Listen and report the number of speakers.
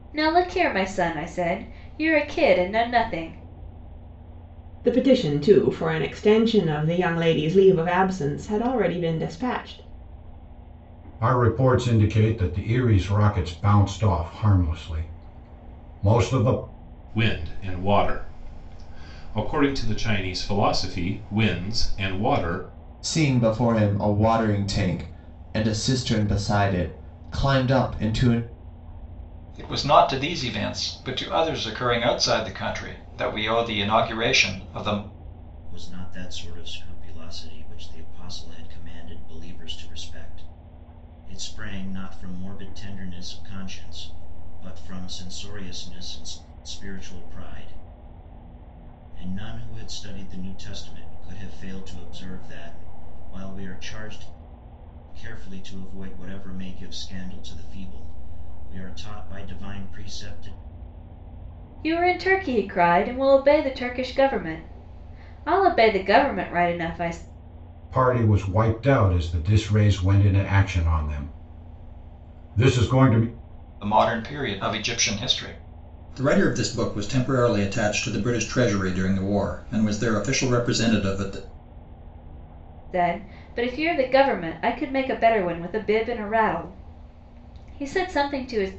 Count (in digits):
7